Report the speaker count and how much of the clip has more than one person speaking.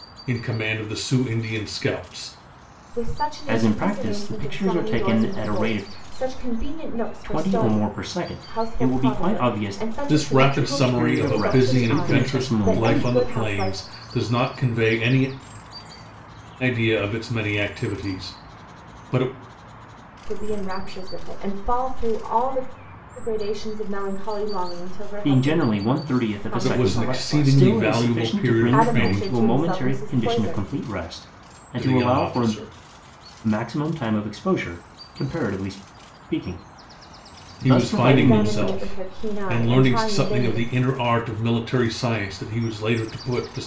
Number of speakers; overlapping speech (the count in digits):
3, about 39%